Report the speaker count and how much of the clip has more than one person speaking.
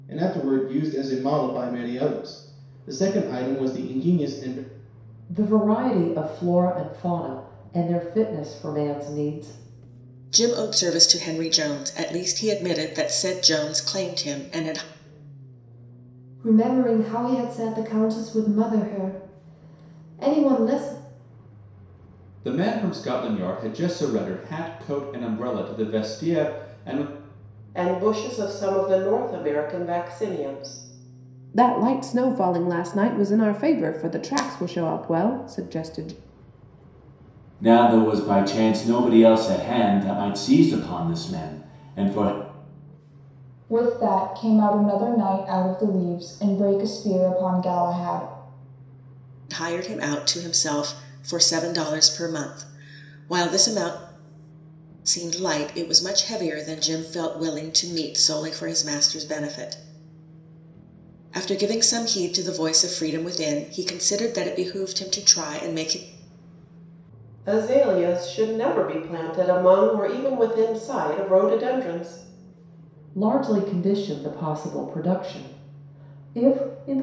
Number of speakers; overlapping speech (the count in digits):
9, no overlap